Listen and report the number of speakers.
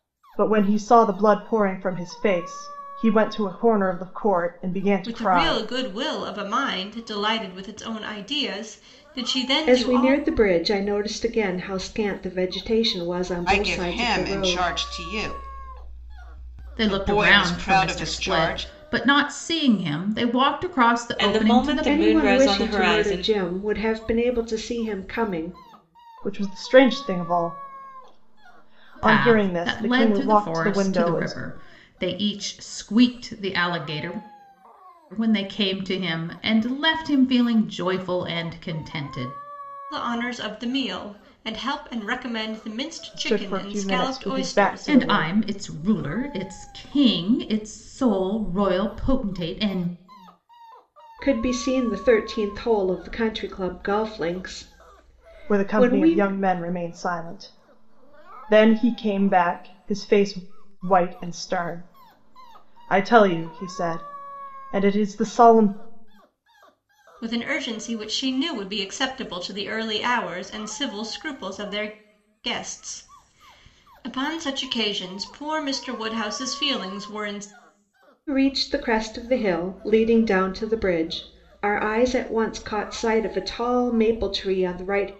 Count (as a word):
six